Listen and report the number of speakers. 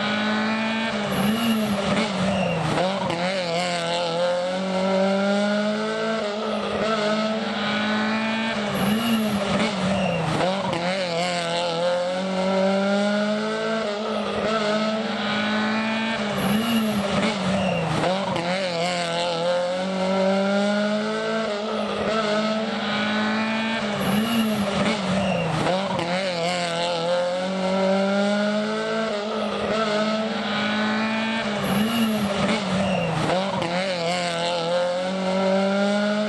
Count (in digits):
0